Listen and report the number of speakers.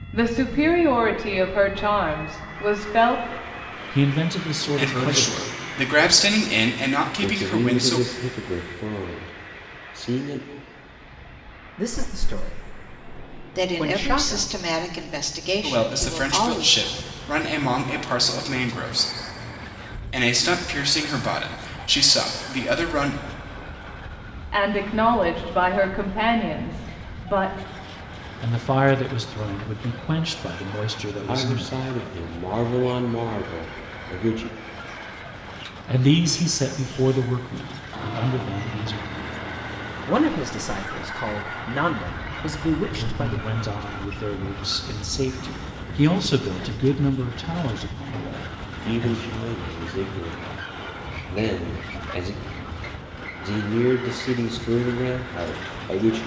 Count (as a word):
six